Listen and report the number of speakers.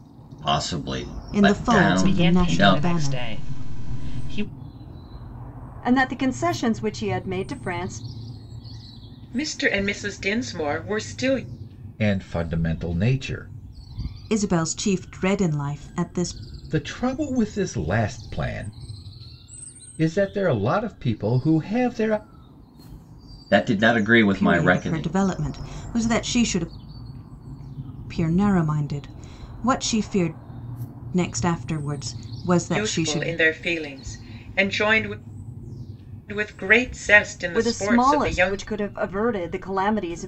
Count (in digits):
6